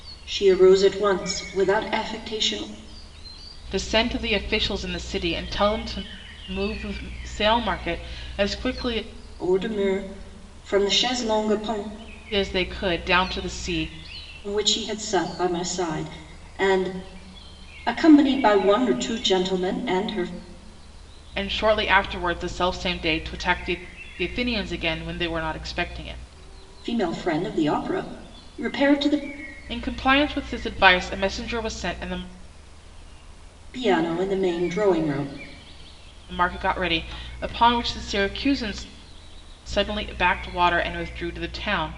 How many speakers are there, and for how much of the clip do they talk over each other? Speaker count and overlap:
two, no overlap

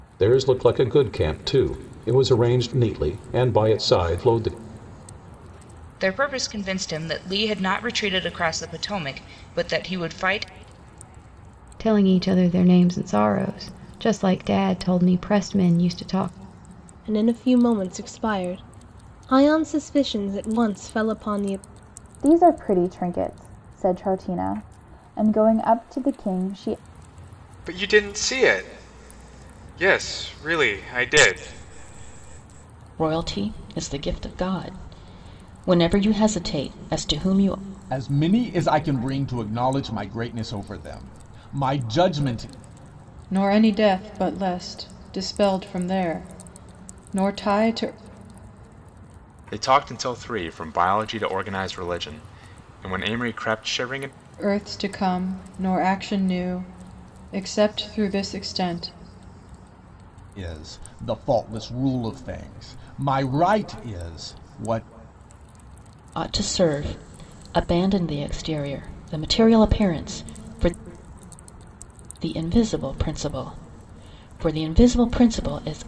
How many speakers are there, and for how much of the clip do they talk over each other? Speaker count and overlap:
ten, no overlap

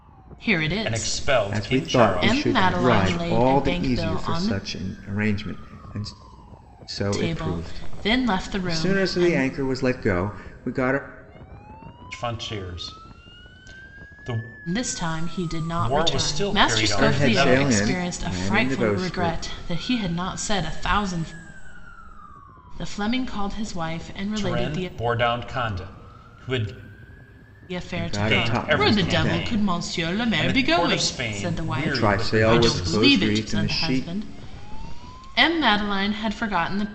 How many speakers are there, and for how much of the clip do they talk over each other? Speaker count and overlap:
three, about 43%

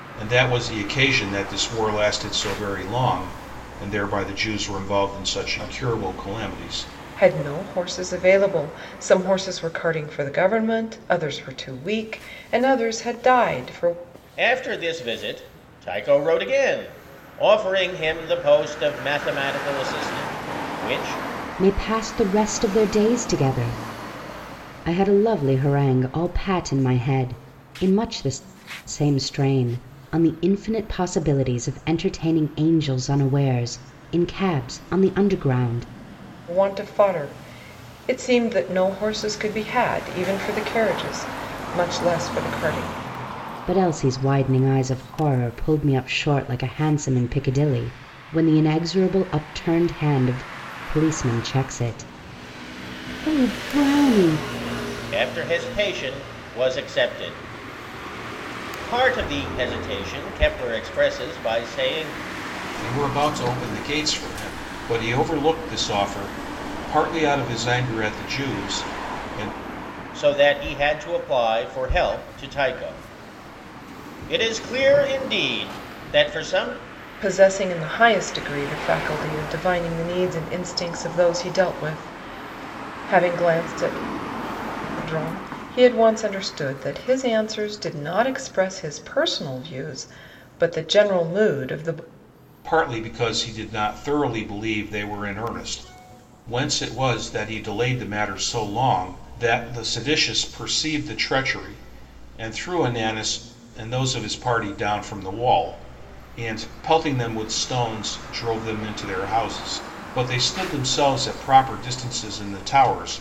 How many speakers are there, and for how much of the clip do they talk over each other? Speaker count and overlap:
four, no overlap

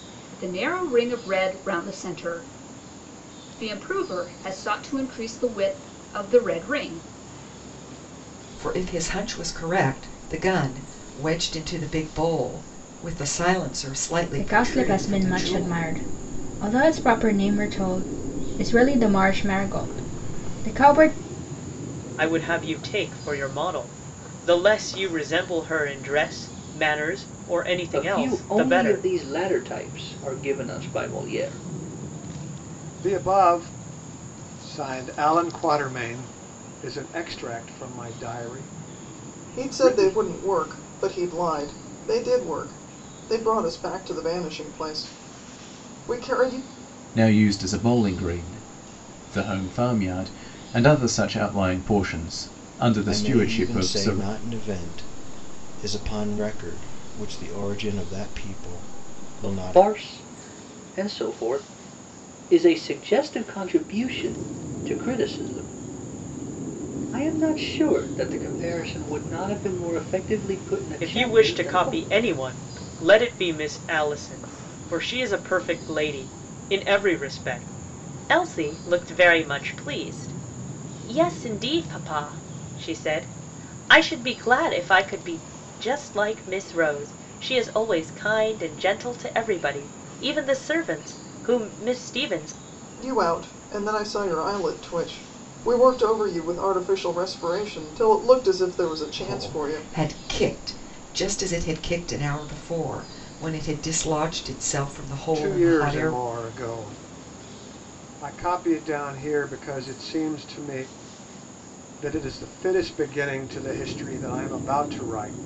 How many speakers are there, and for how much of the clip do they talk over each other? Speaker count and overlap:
nine, about 7%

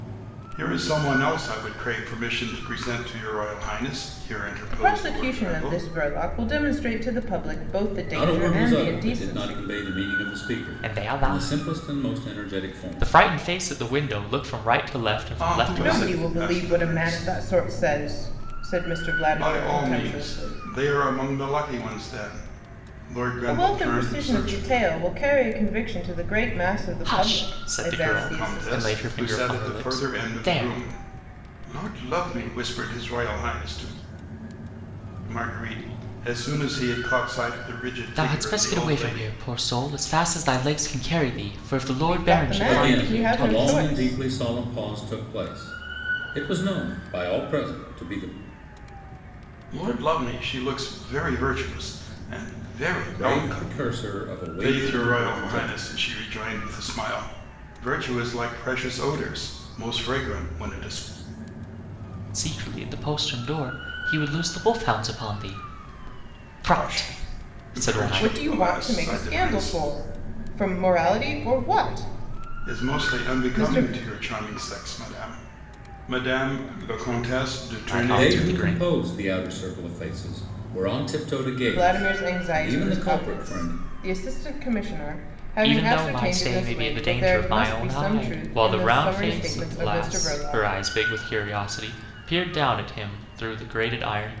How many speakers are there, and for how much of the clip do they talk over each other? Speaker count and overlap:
four, about 35%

